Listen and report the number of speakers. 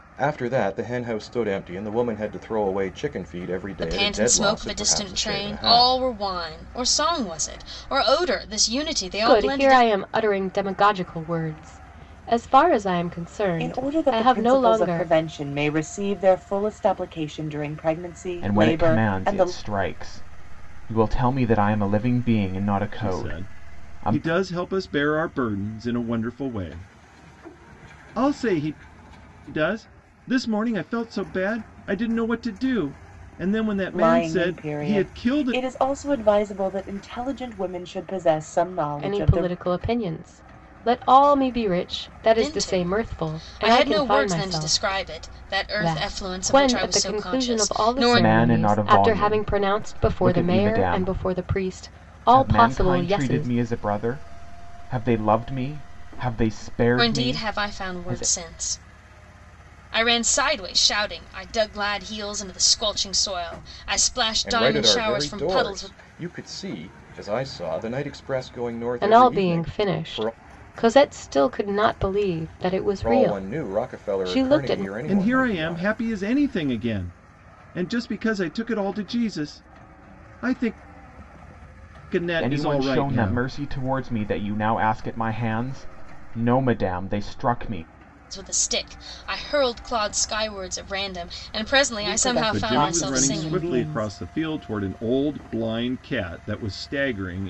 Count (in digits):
6